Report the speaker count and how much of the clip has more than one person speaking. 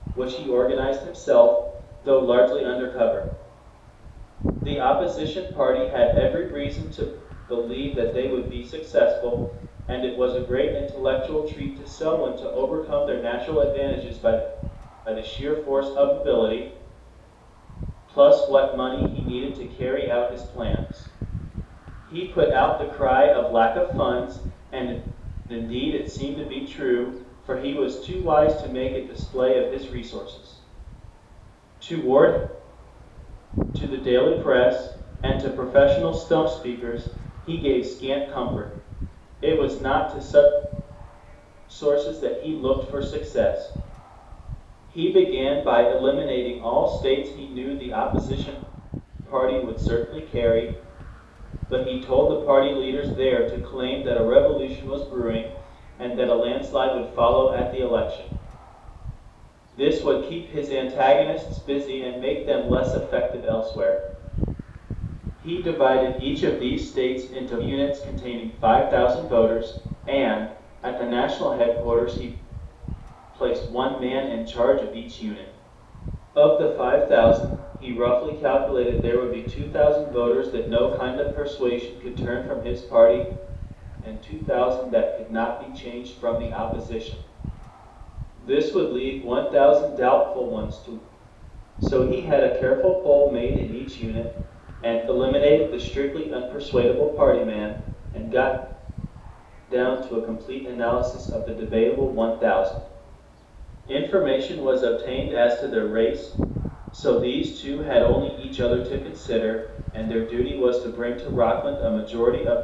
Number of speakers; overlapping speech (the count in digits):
1, no overlap